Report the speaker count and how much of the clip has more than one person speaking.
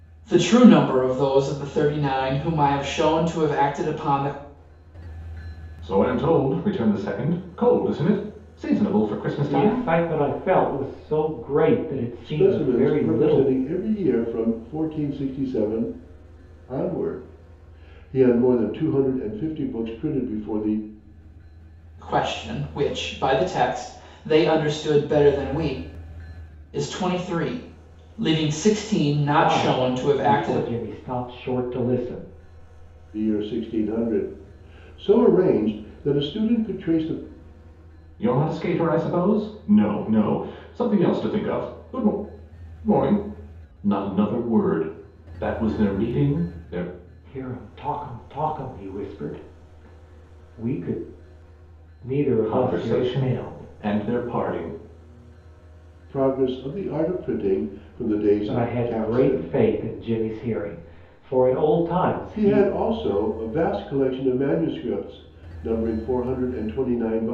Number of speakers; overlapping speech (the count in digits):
4, about 9%